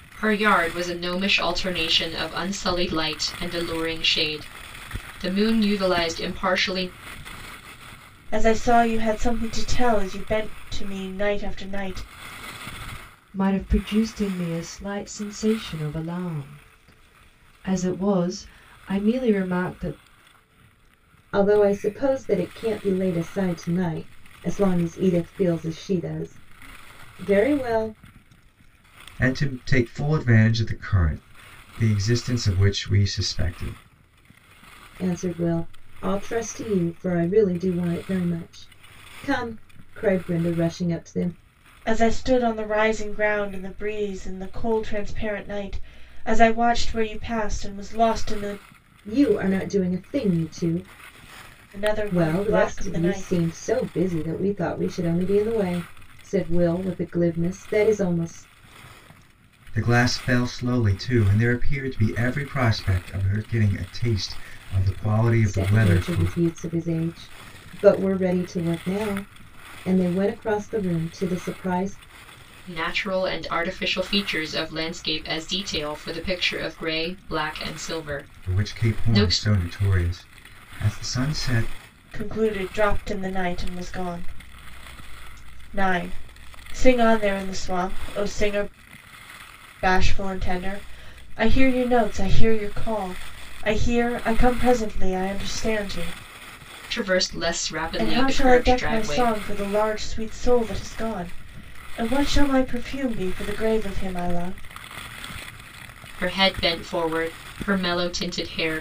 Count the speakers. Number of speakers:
5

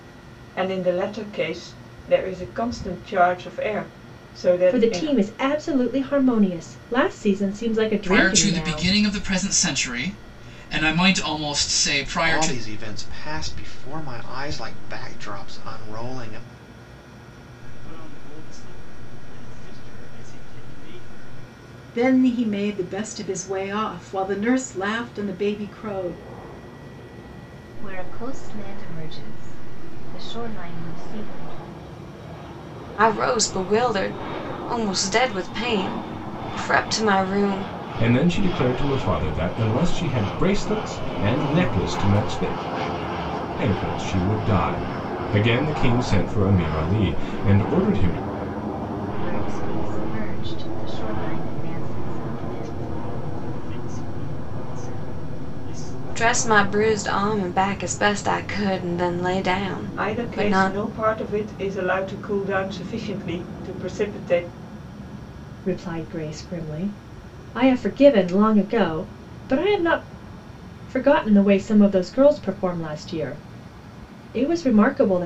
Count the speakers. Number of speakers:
9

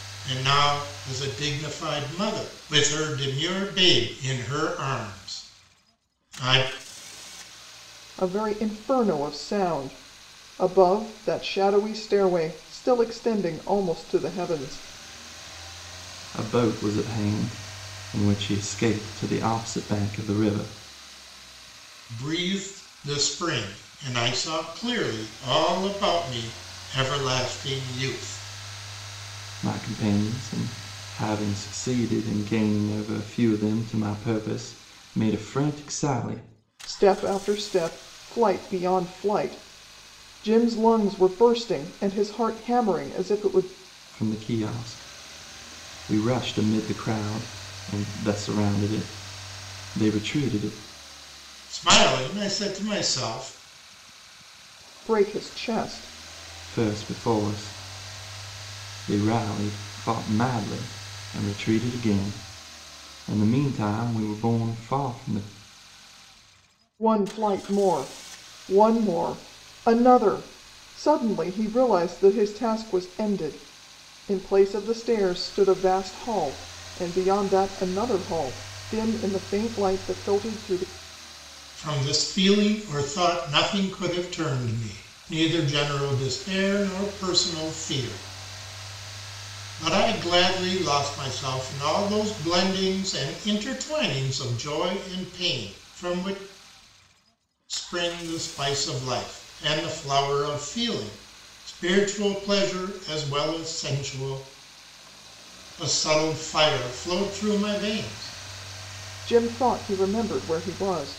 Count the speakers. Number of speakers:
3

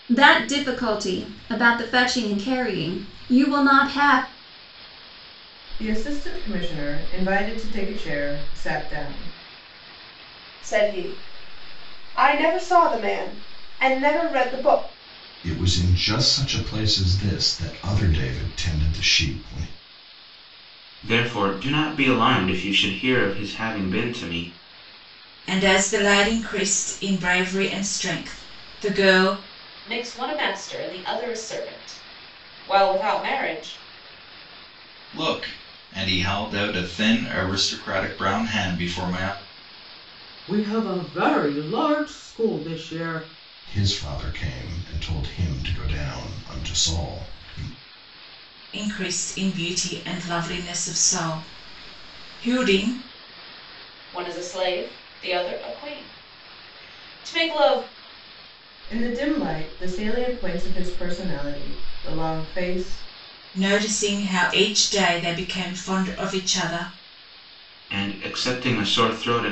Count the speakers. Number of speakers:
9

